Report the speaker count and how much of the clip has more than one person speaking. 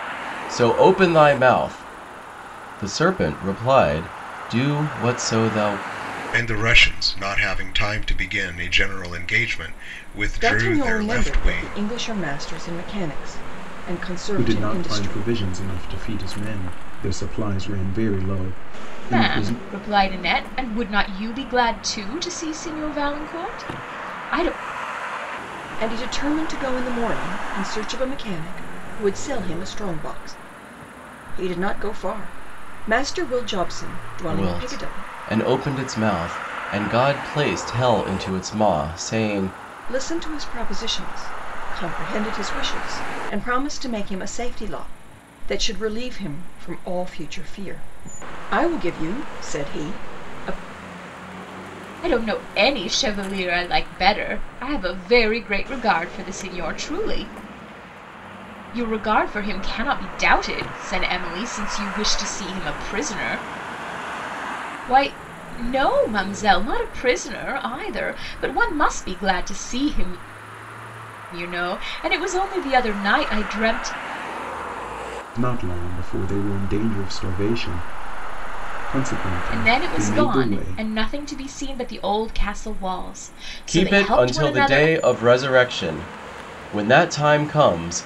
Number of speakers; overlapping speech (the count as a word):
five, about 7%